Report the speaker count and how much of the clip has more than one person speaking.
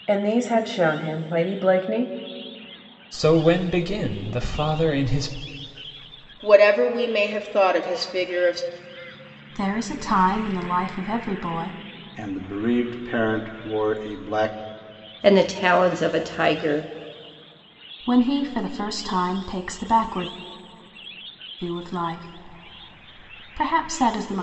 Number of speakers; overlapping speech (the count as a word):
six, no overlap